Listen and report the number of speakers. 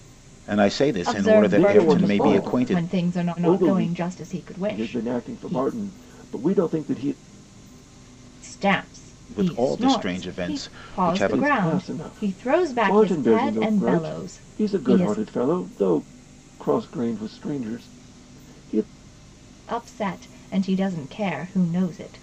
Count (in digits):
3